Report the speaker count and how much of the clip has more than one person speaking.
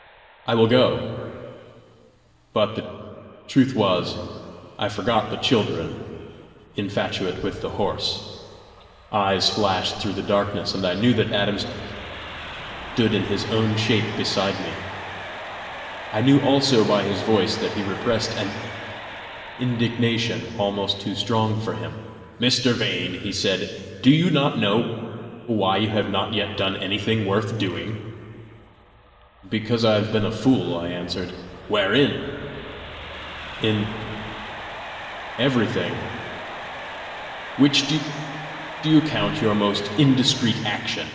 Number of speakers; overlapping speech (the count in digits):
1, no overlap